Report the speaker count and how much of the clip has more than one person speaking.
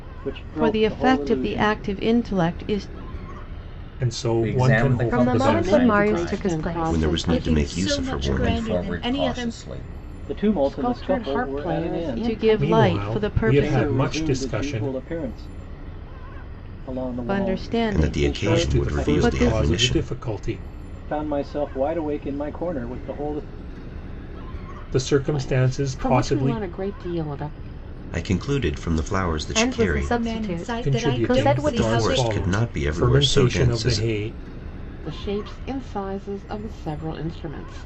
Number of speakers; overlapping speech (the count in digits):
8, about 51%